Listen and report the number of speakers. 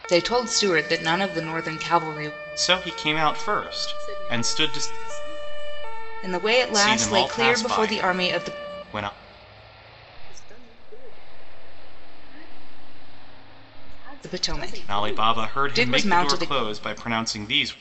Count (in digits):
3